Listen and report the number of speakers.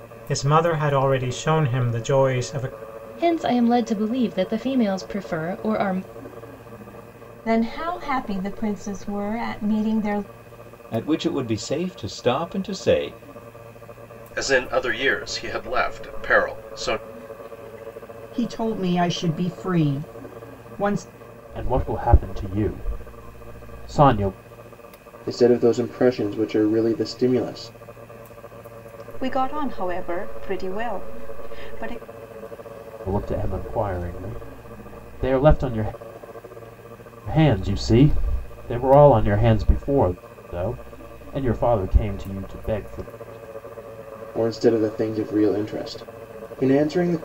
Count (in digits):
9